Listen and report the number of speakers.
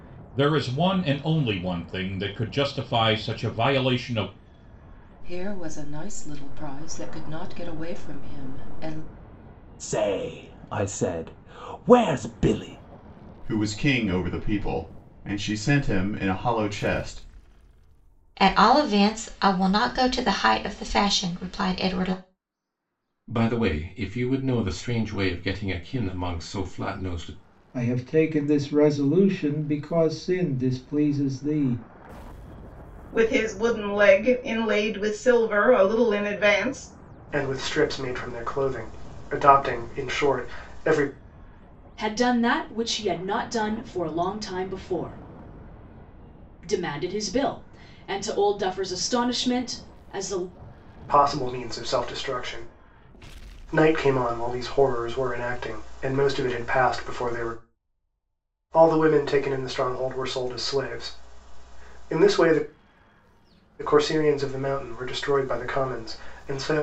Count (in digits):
10